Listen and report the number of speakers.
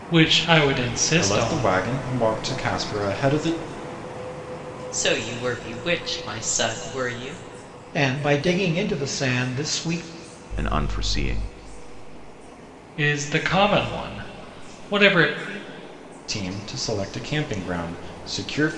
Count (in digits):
5